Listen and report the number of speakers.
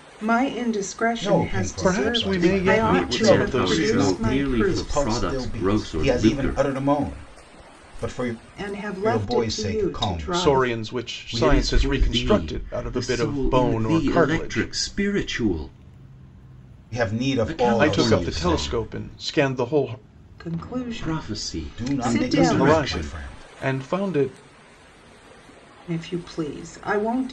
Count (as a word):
four